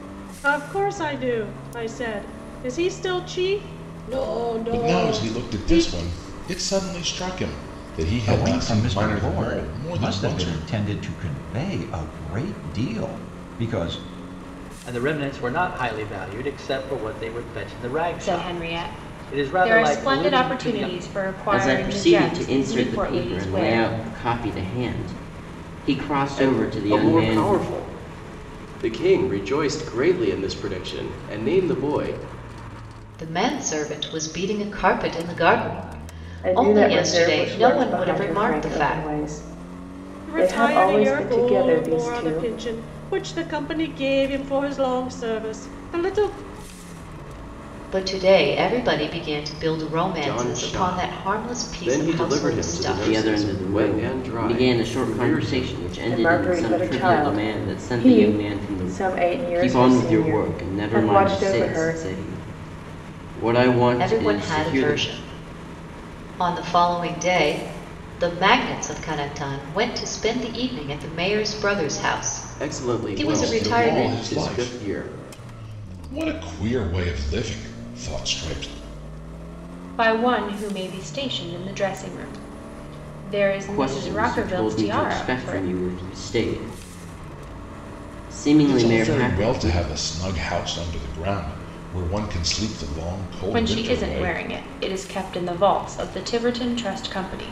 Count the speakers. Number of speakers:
9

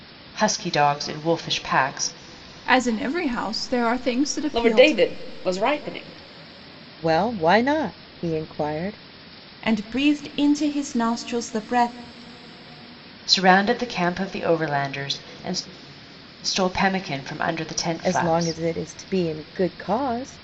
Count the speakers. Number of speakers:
5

